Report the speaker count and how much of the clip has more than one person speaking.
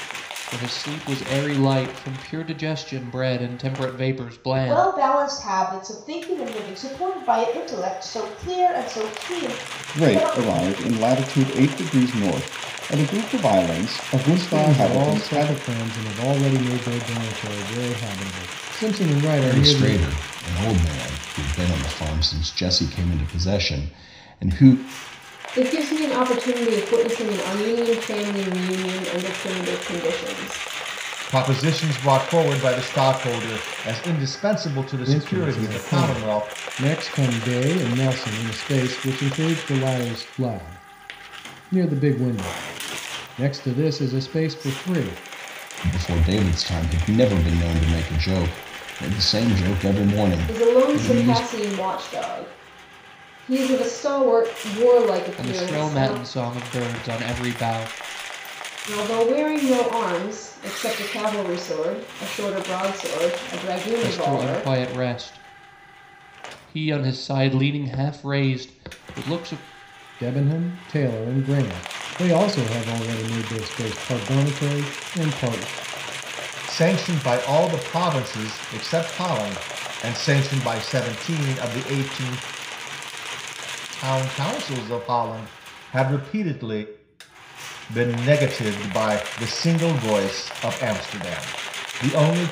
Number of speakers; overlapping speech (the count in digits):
7, about 8%